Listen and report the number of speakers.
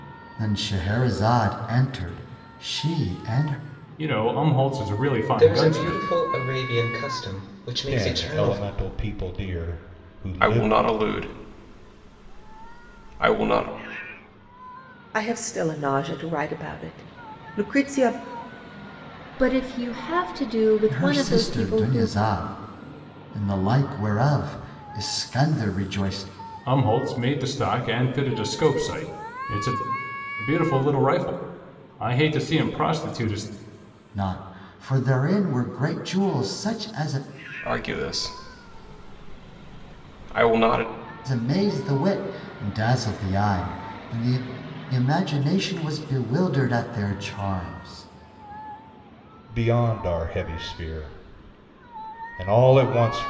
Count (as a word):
seven